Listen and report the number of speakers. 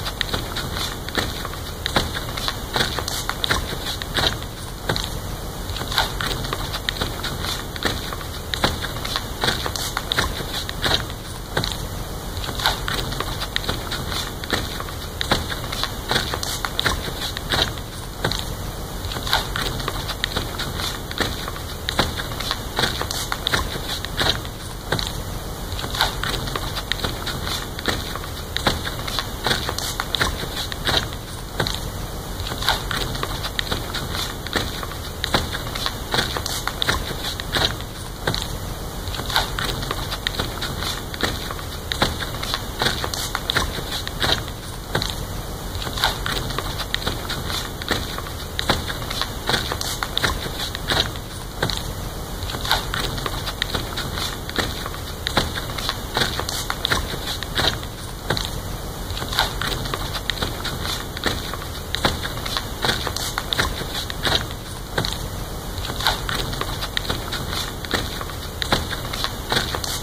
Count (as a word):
zero